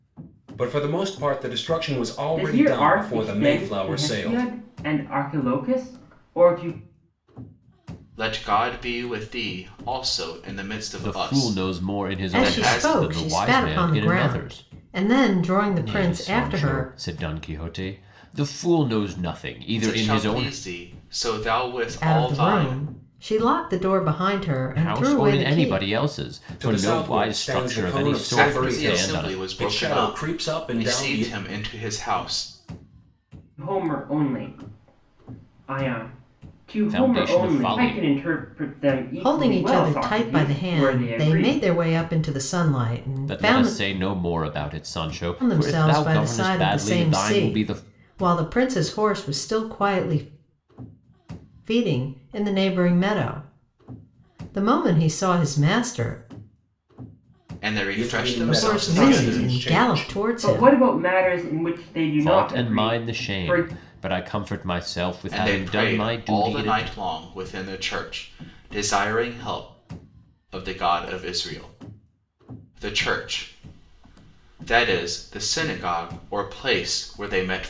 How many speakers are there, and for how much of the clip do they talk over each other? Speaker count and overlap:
five, about 34%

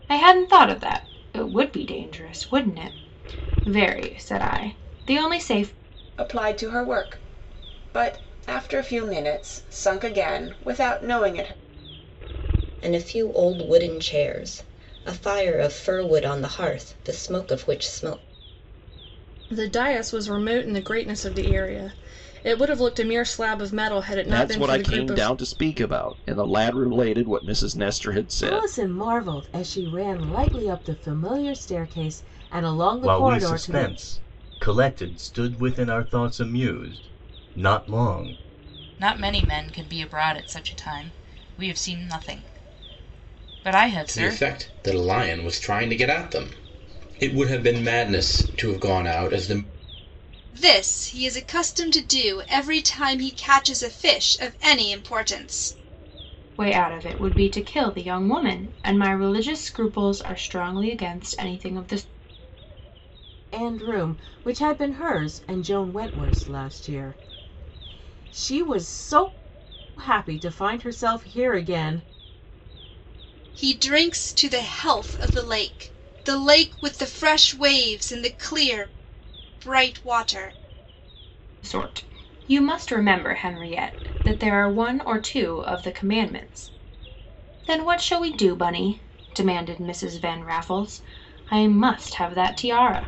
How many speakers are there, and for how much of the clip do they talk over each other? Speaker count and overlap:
ten, about 3%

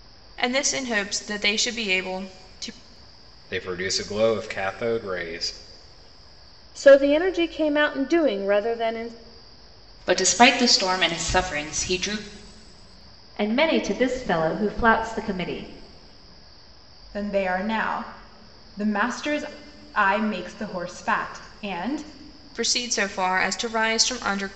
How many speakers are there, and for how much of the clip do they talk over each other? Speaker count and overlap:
six, no overlap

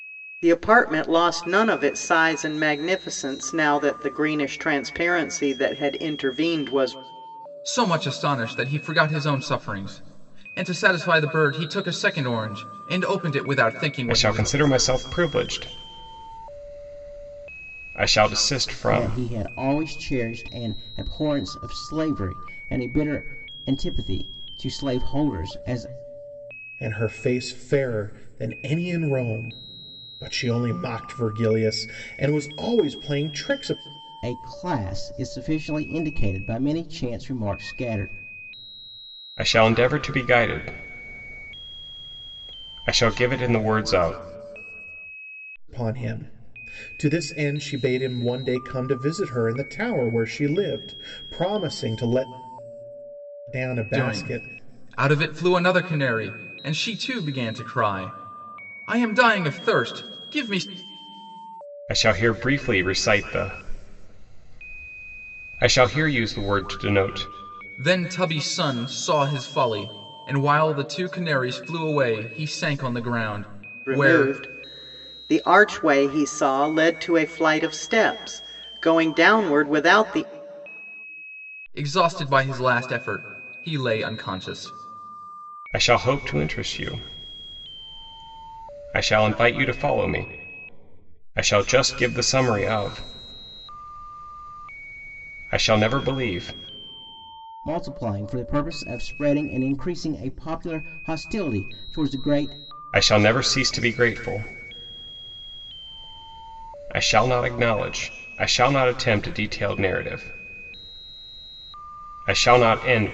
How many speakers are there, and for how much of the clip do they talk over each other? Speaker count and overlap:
five, about 2%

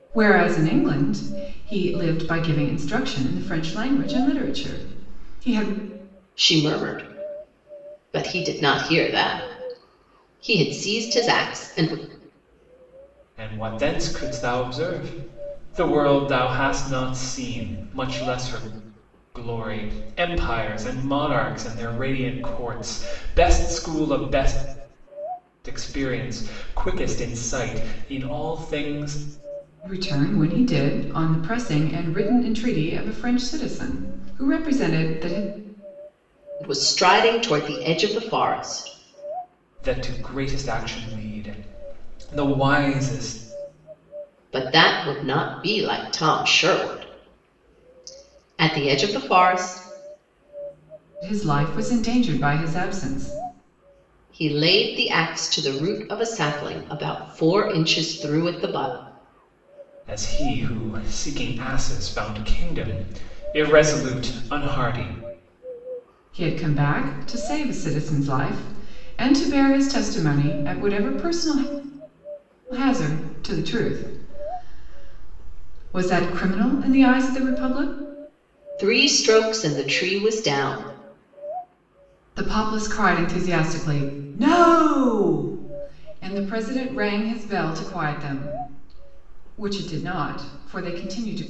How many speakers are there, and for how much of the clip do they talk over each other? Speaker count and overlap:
three, no overlap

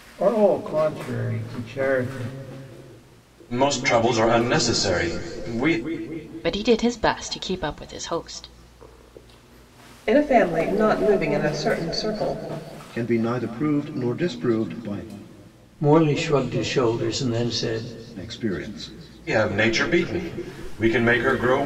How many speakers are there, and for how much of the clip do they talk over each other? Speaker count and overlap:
six, no overlap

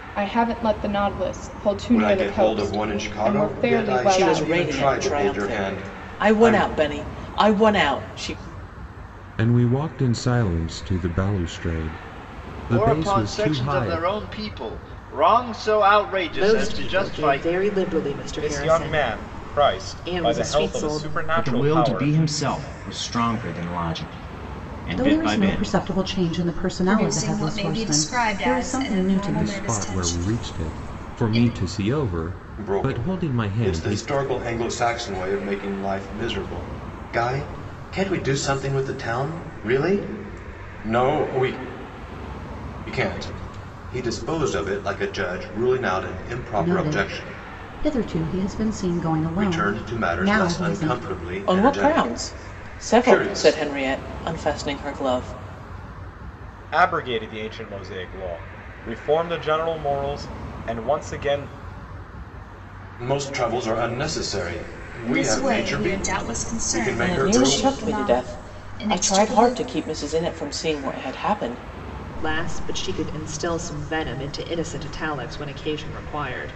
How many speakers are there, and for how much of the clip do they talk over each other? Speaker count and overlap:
ten, about 35%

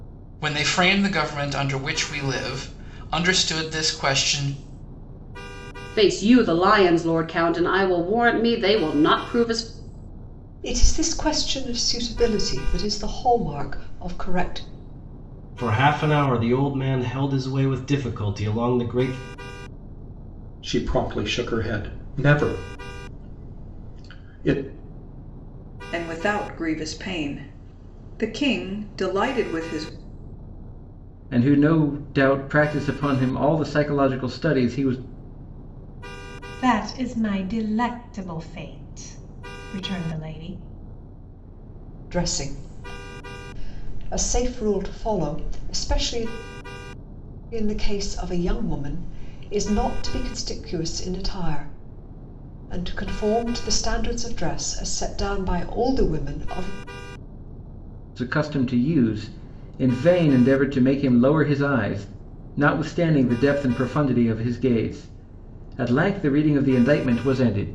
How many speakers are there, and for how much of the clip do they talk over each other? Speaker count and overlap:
eight, no overlap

